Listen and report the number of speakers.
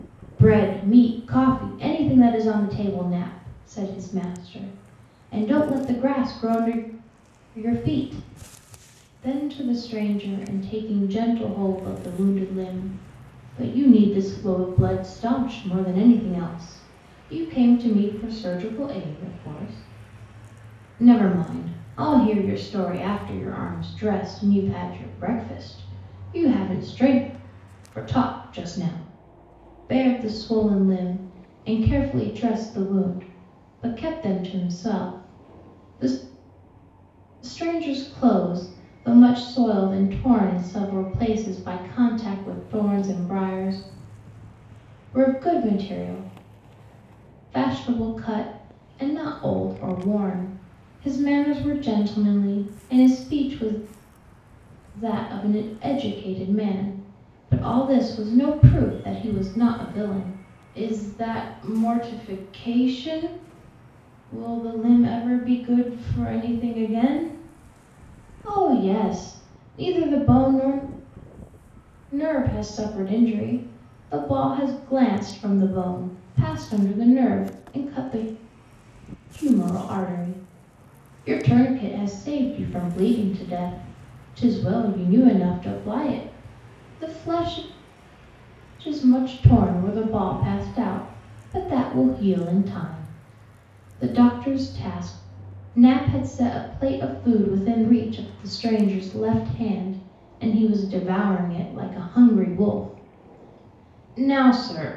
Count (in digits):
1